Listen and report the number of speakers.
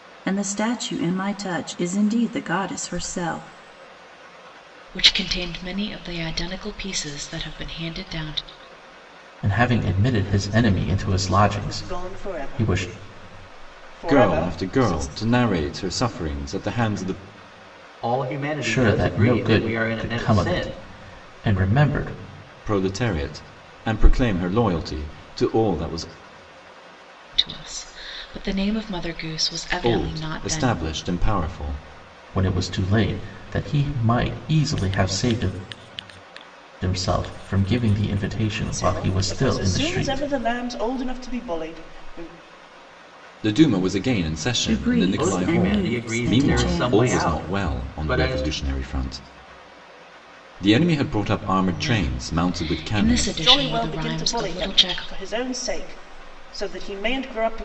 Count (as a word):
six